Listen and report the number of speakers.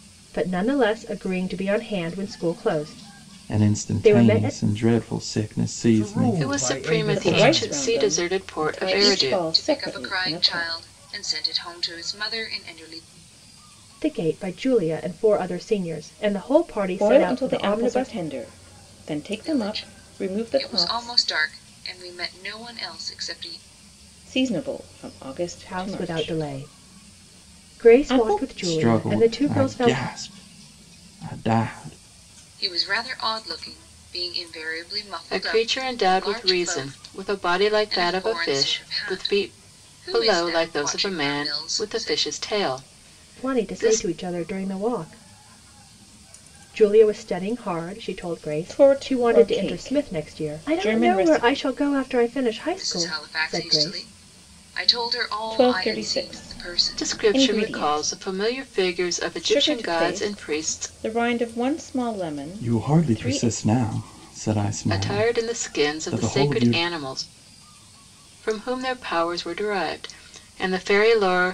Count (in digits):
6